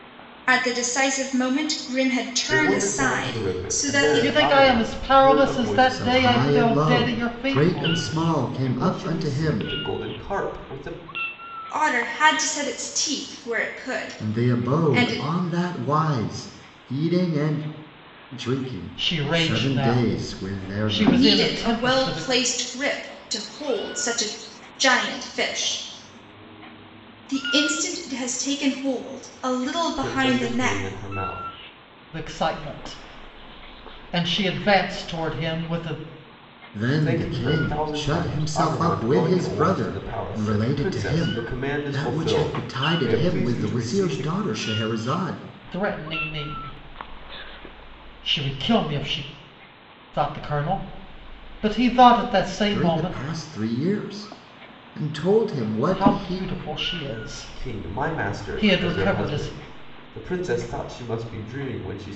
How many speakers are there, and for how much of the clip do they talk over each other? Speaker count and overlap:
4, about 37%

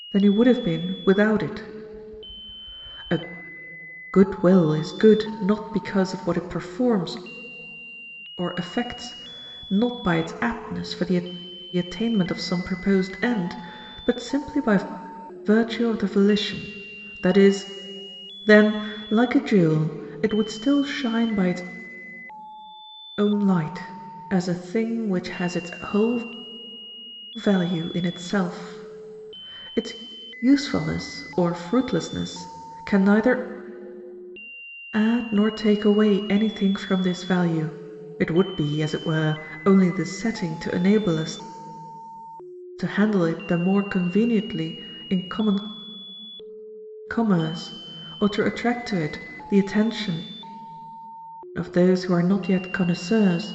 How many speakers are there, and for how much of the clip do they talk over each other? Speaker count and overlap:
1, no overlap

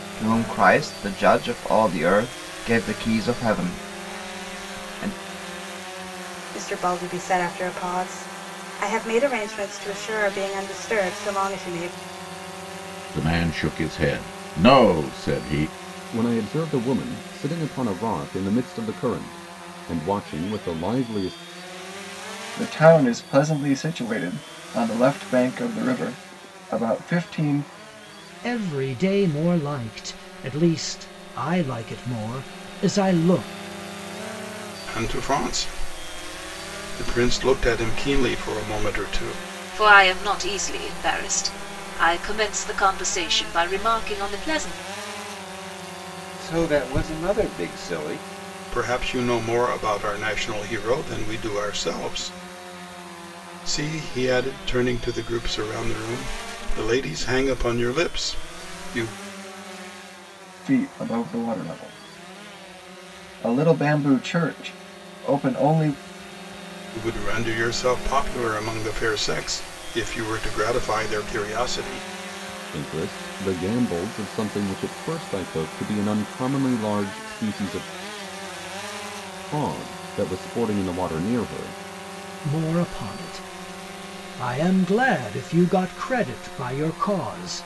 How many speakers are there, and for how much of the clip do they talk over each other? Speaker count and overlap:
9, no overlap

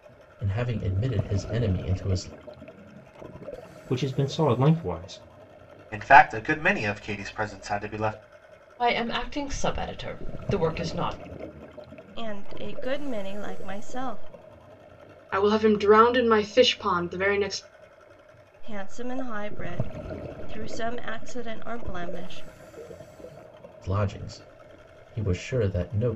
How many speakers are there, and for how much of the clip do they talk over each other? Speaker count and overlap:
6, no overlap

